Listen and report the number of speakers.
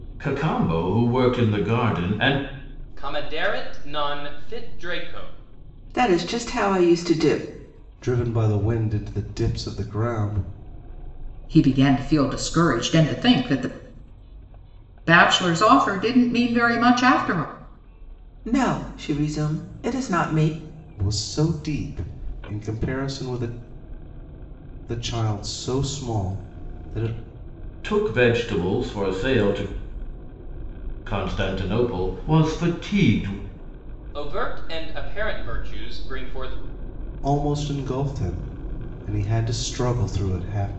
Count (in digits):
5